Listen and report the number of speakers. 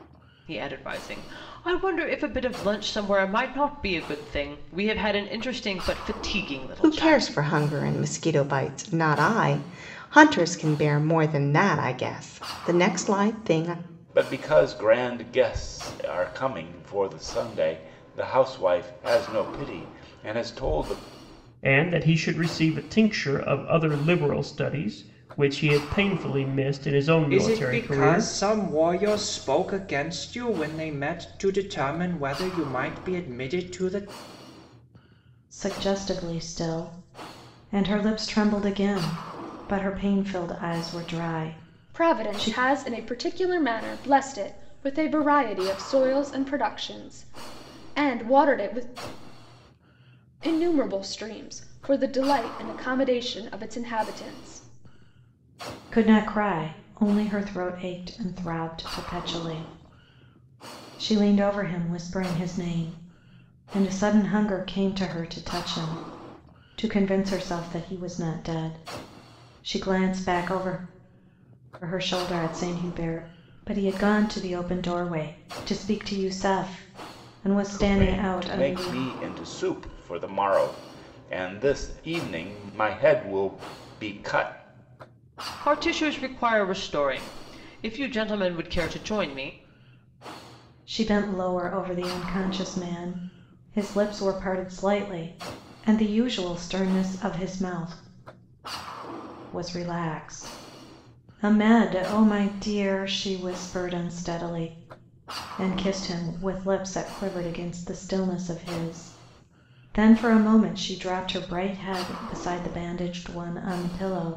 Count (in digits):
7